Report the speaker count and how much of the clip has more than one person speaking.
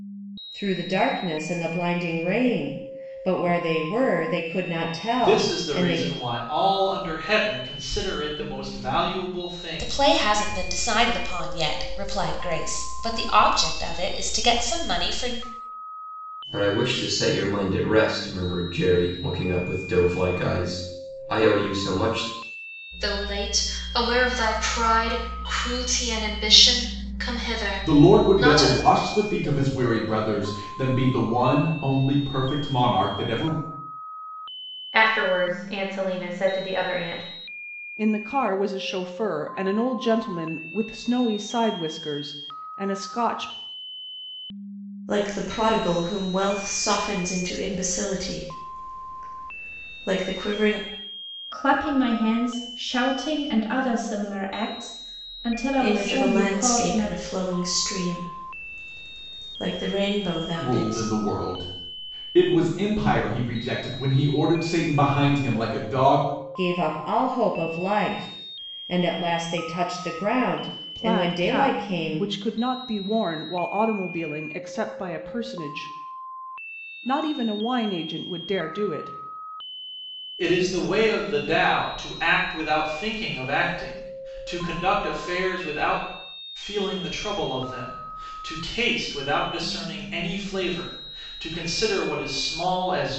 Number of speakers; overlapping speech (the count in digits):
10, about 6%